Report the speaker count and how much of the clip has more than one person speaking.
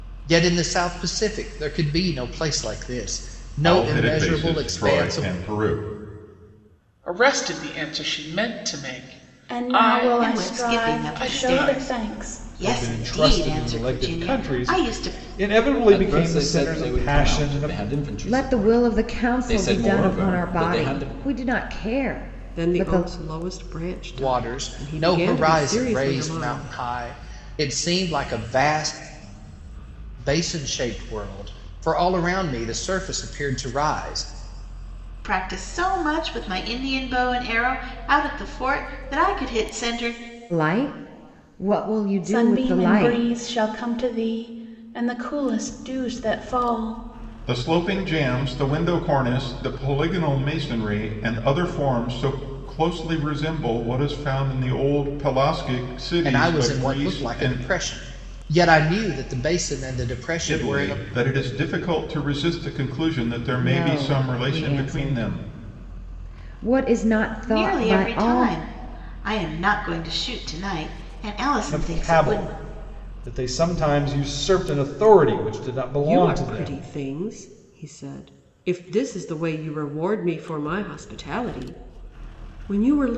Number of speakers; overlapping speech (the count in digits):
9, about 28%